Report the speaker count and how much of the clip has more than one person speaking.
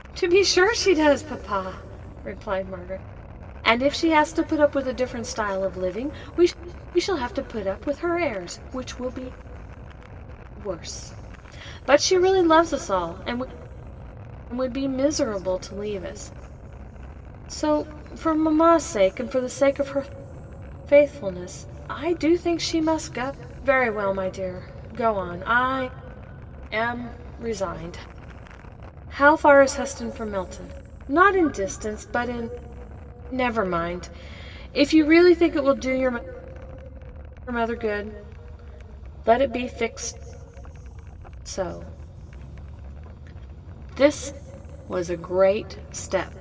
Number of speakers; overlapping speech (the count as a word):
one, no overlap